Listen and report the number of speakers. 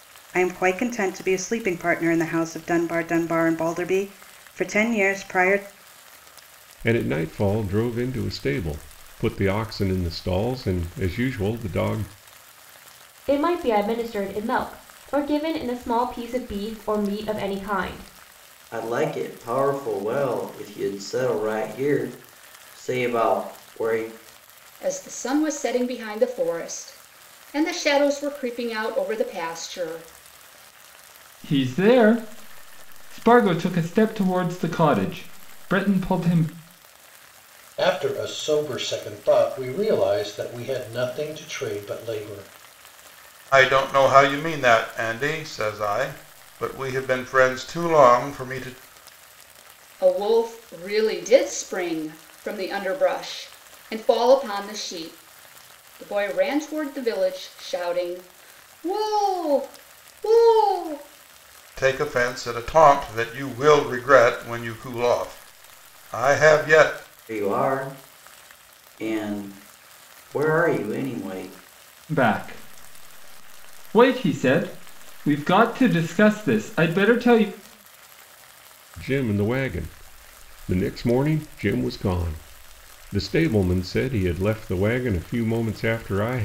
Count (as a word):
eight